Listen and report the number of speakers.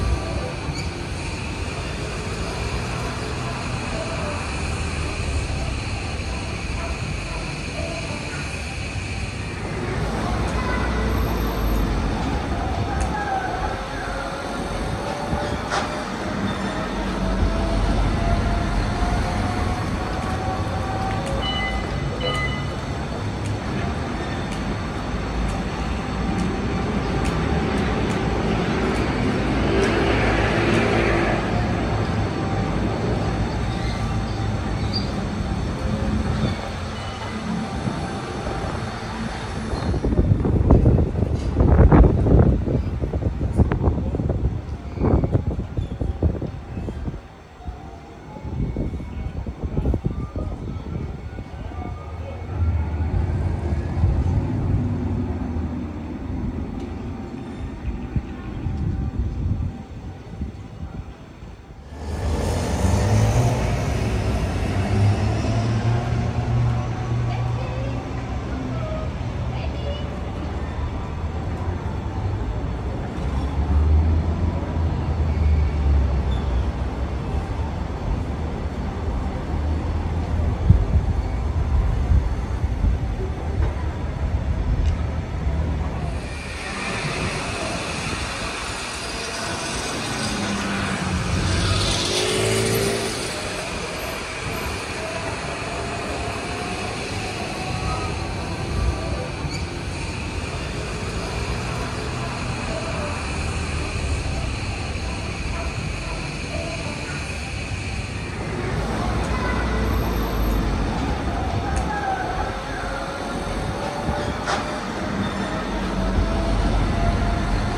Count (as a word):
zero